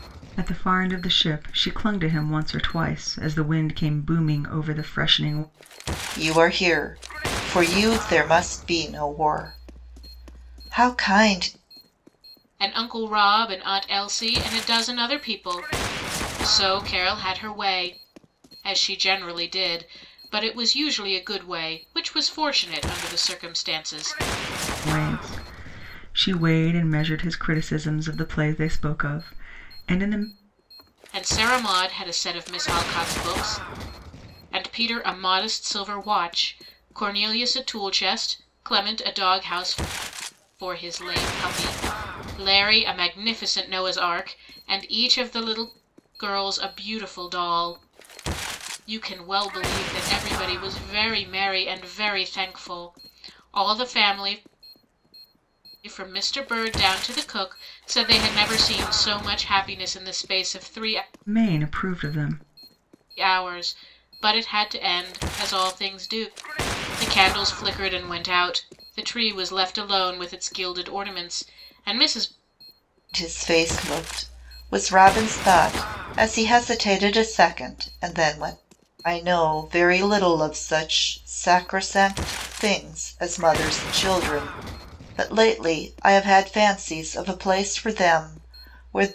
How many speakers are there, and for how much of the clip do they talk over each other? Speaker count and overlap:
3, no overlap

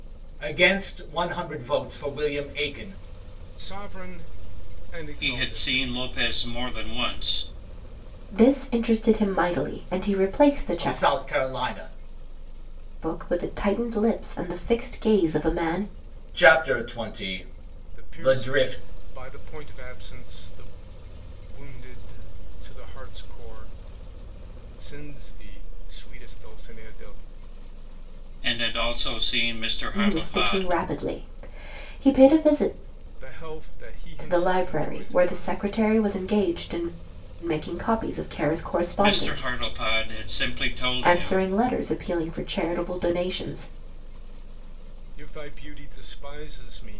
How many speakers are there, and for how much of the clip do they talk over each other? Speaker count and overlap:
4, about 12%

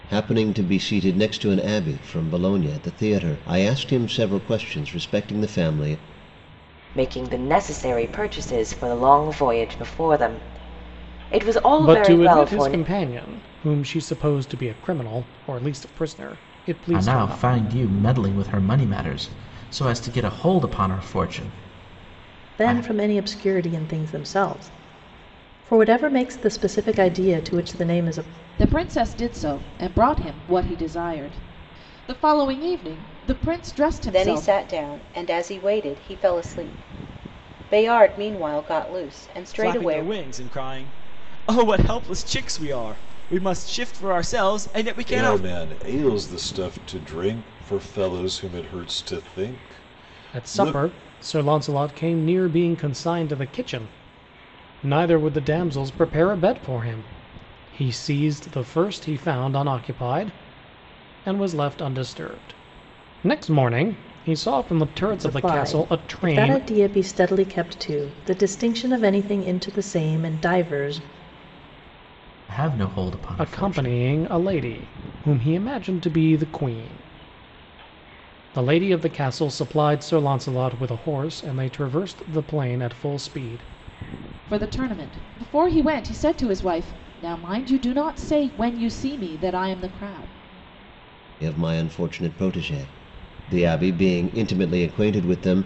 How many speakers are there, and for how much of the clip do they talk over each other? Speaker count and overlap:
9, about 6%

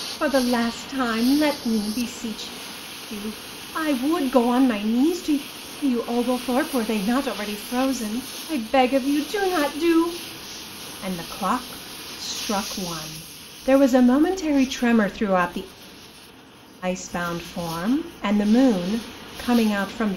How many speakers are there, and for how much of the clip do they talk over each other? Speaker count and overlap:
1, no overlap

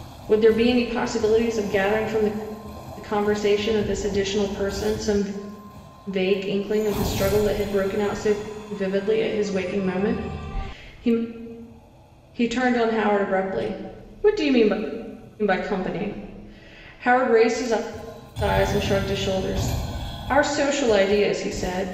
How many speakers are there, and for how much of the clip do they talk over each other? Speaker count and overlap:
1, no overlap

